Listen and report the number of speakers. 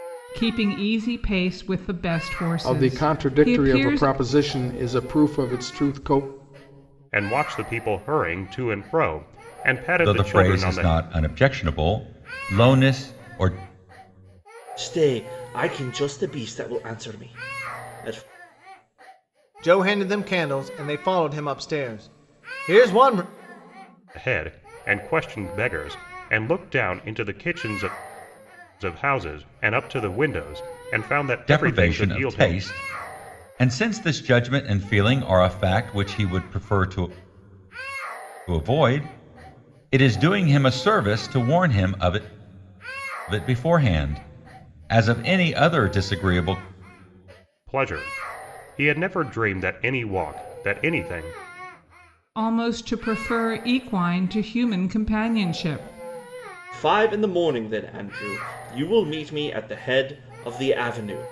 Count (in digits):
6